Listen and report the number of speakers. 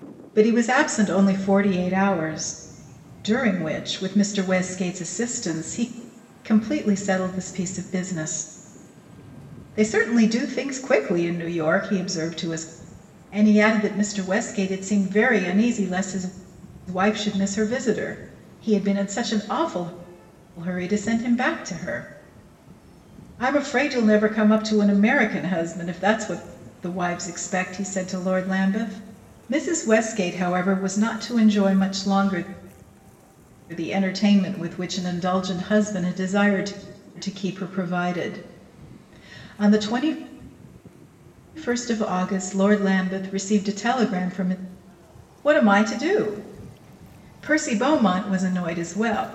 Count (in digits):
1